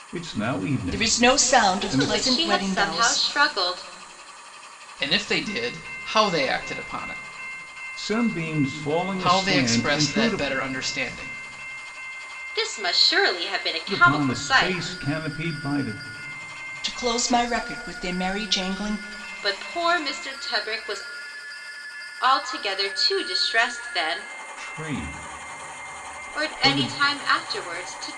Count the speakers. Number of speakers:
4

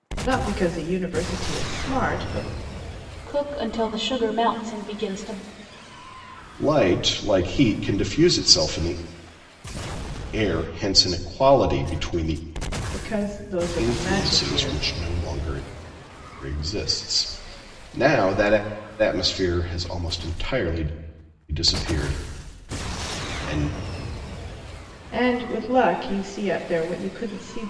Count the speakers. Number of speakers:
3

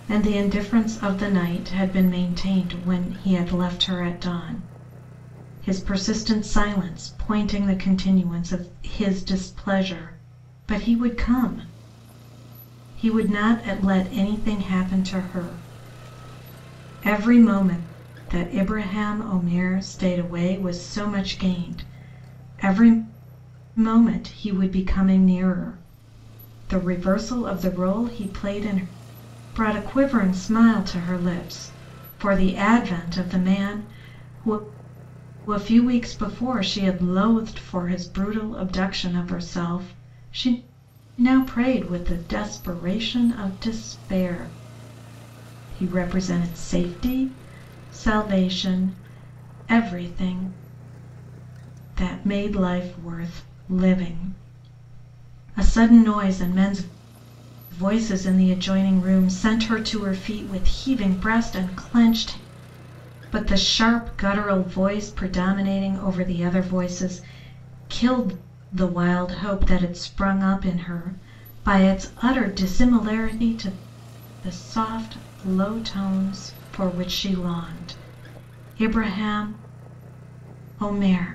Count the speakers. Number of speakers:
1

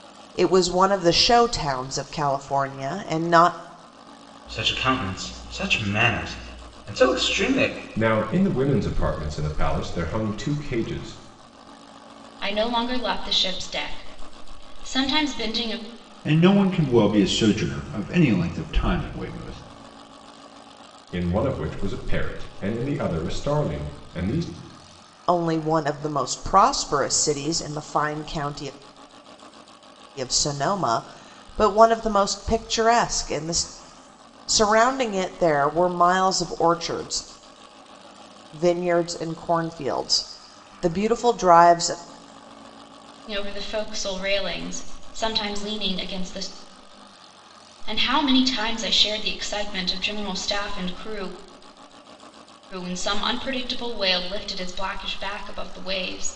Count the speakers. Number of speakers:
5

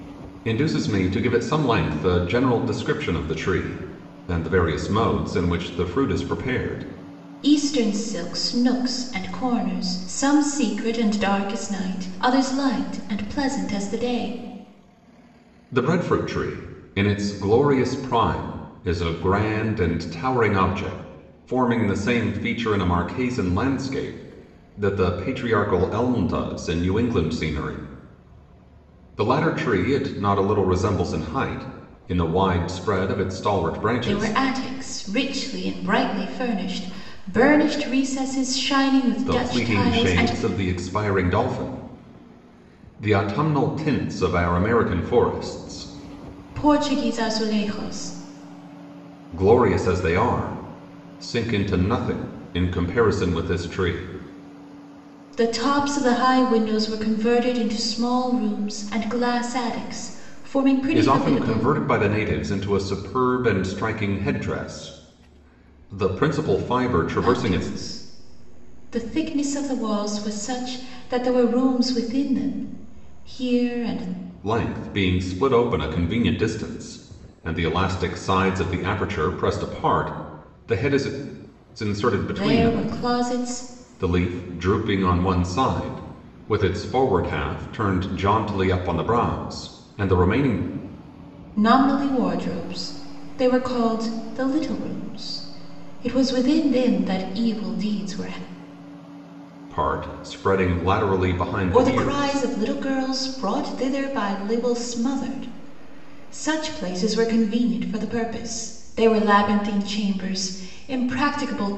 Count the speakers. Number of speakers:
2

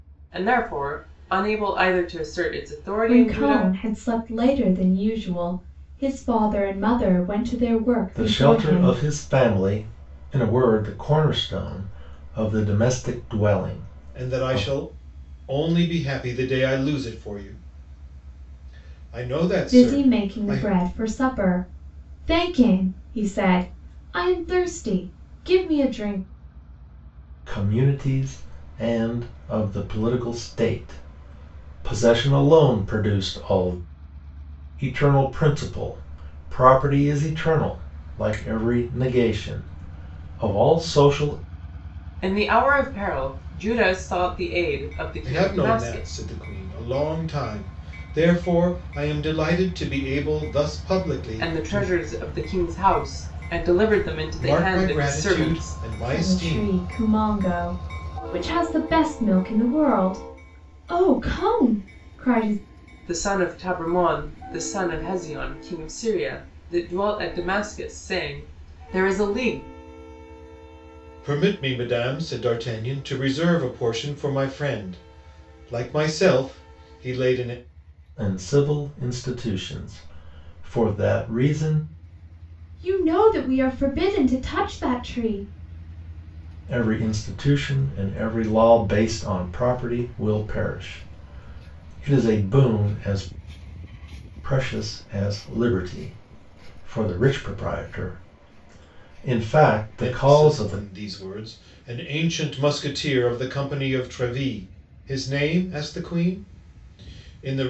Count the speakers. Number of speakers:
4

